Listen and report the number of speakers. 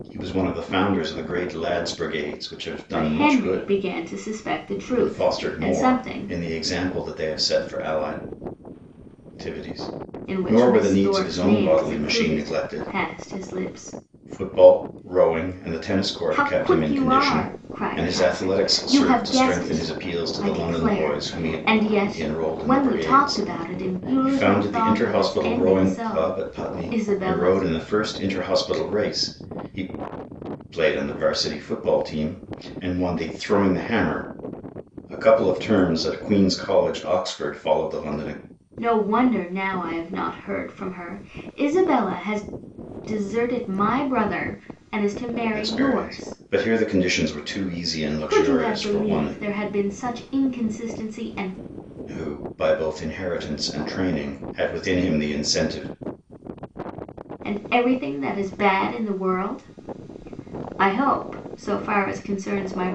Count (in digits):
2